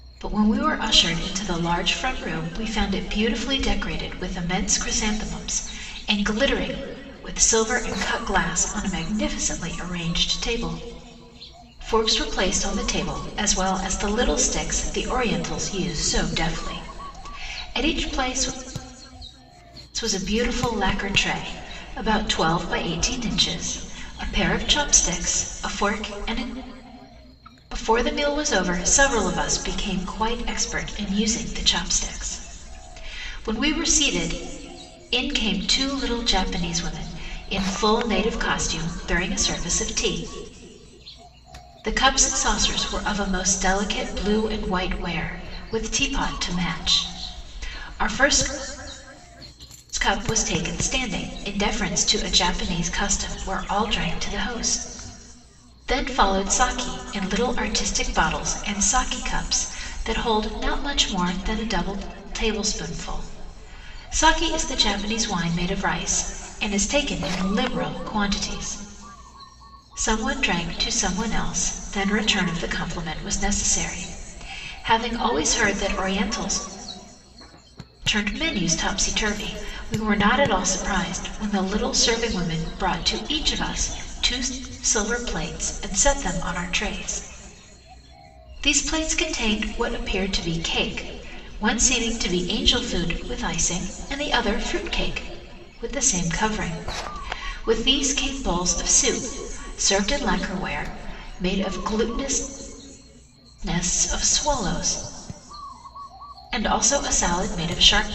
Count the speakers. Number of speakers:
1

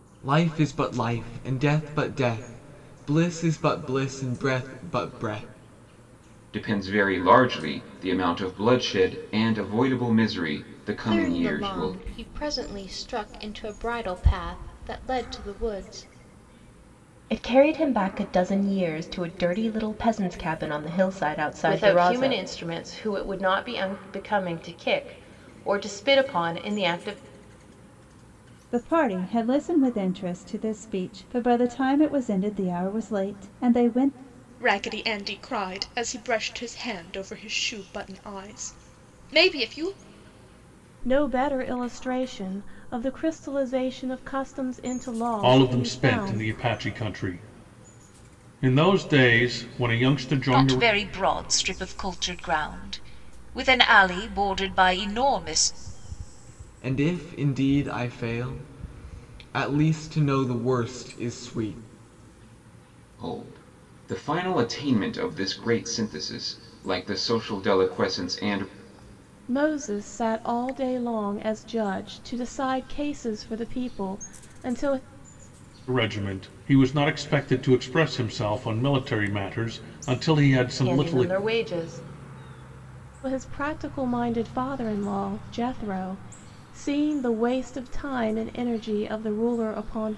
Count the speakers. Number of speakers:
10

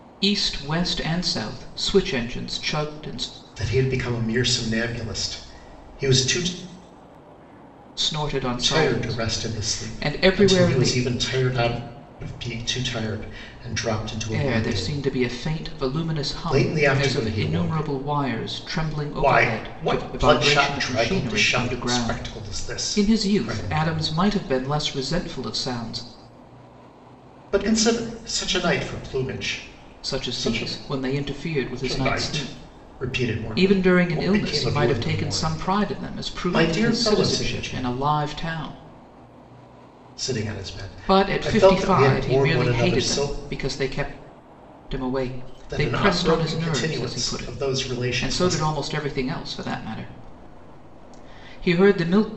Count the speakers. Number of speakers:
2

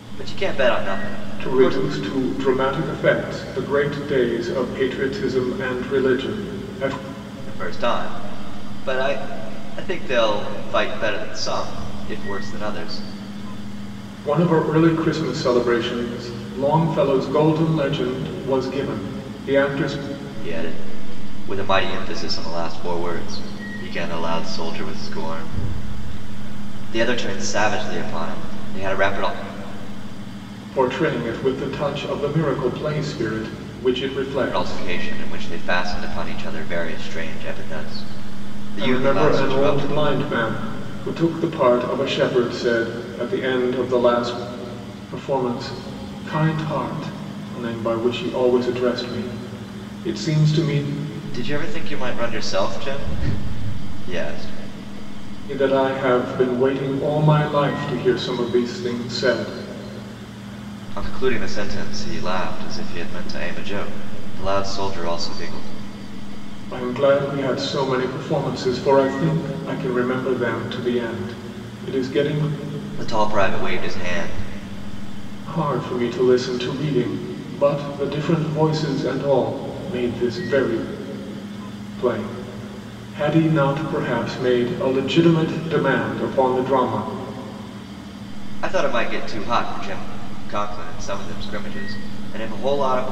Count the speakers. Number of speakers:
2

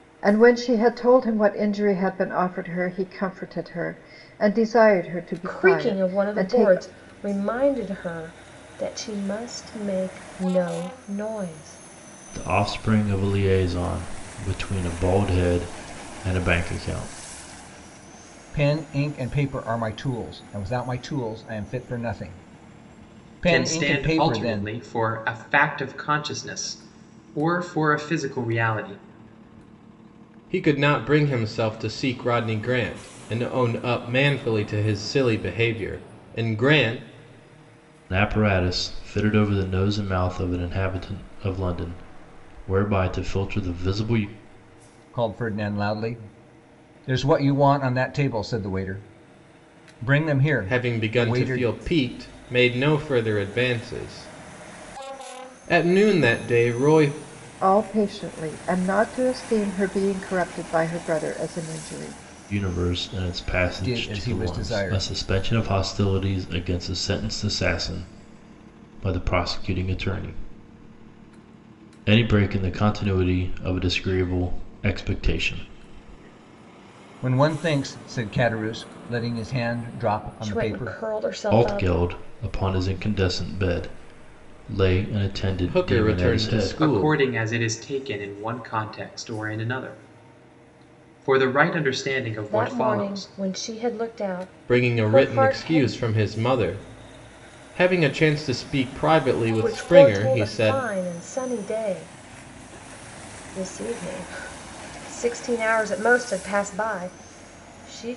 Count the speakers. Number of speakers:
6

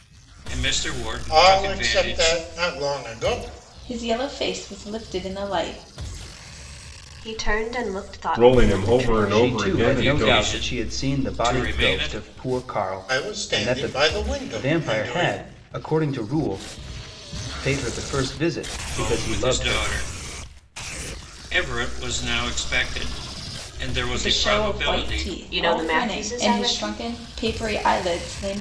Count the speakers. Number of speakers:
6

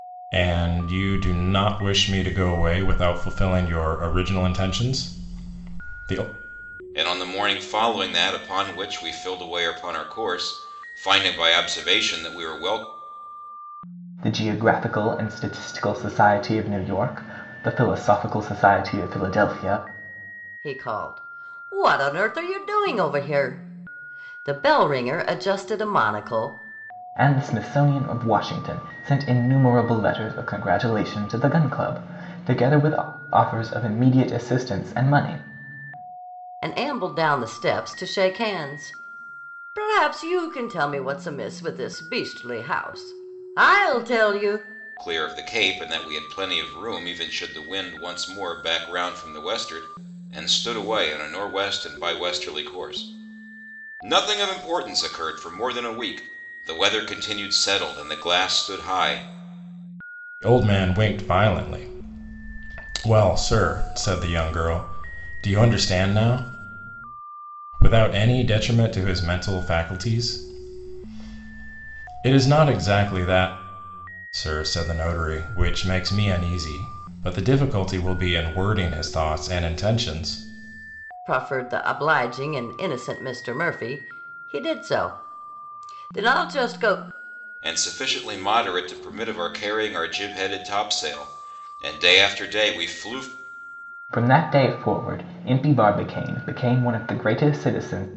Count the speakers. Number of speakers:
4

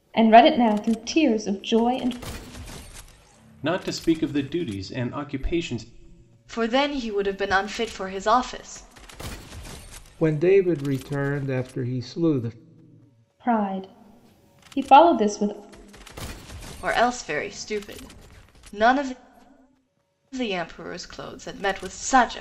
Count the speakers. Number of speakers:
4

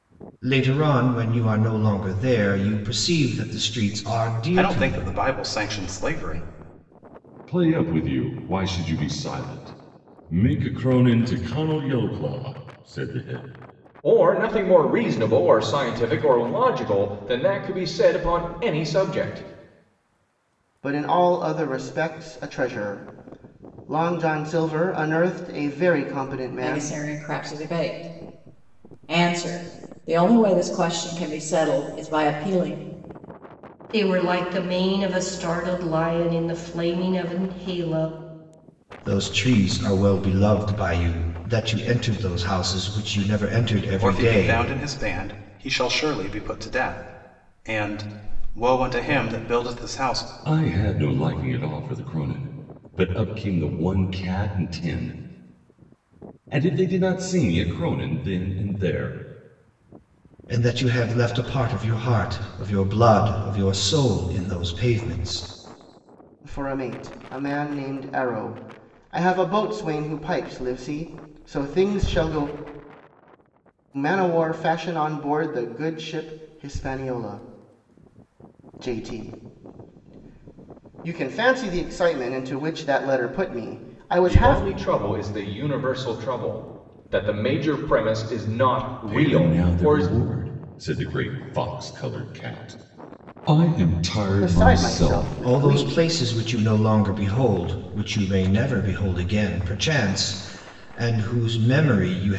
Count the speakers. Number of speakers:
7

